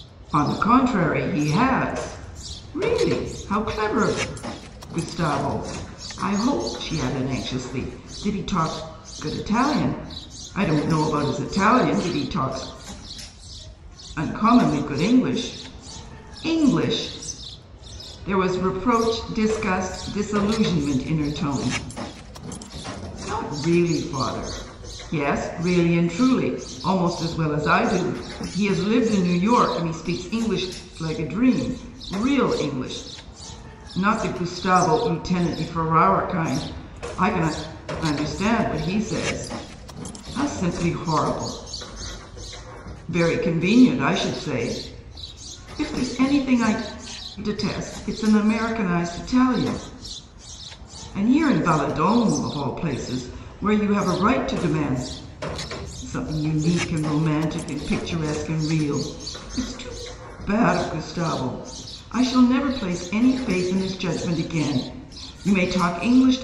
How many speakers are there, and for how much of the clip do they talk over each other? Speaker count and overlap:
1, no overlap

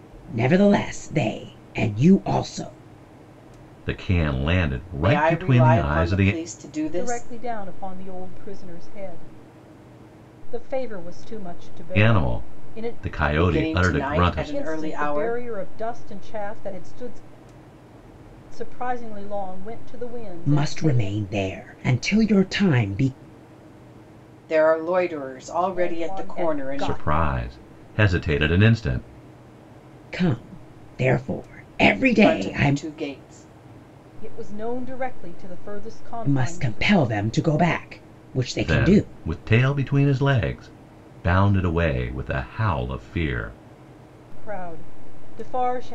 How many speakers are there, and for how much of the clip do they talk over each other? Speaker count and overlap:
4, about 19%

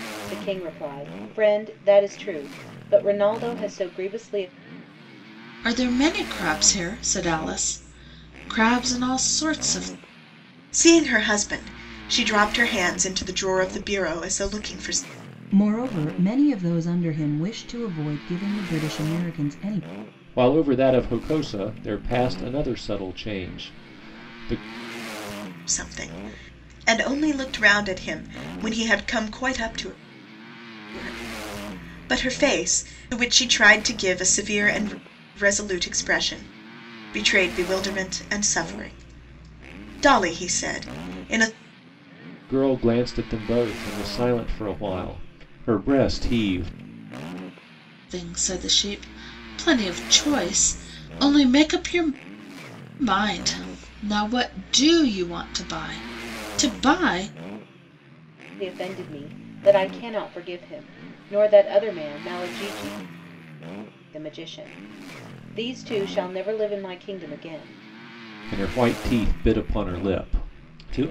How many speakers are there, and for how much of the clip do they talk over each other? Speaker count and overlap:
5, no overlap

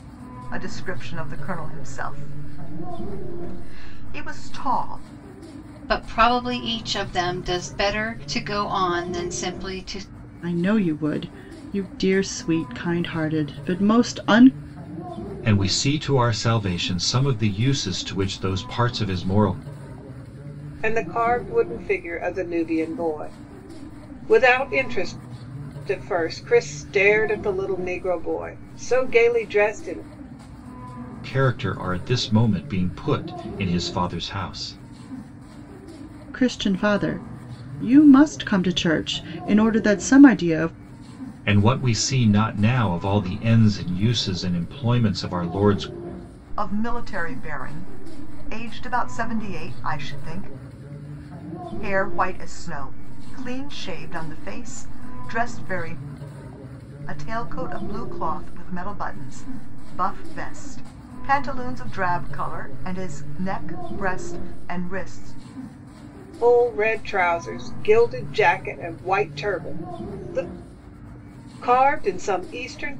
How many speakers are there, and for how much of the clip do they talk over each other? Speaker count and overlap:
5, no overlap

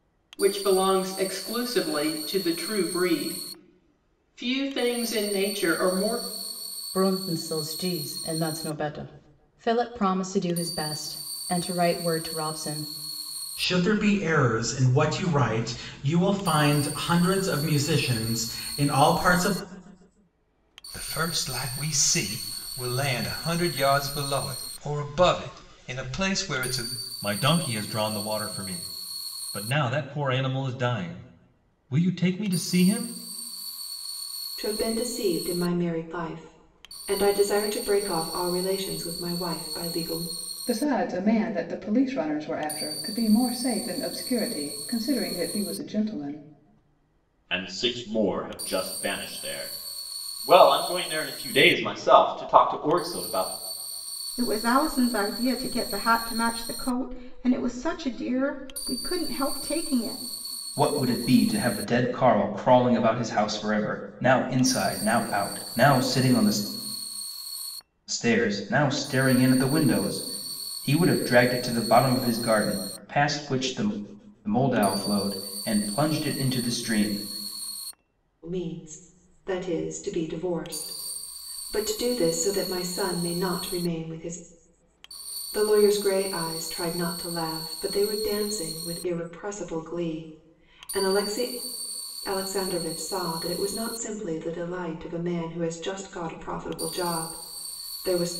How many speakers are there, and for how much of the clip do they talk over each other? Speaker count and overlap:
10, no overlap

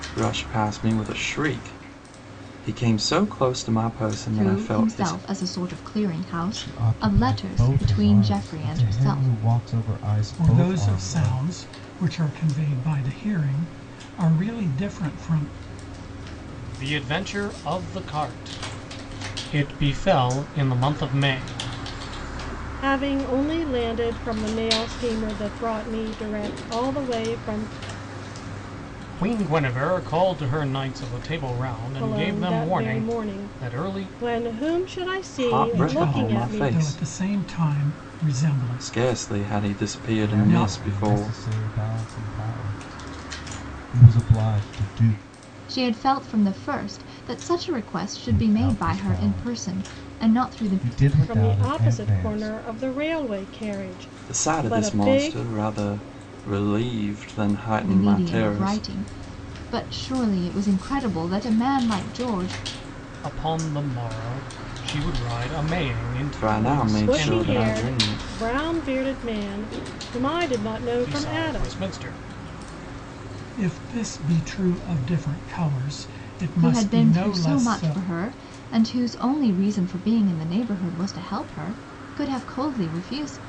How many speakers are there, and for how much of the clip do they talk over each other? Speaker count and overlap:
6, about 26%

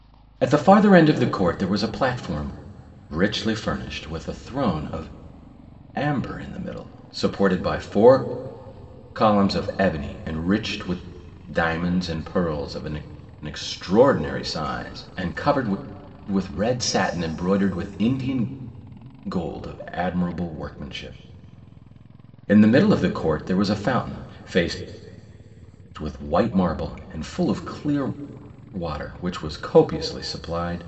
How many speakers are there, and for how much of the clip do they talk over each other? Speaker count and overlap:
1, no overlap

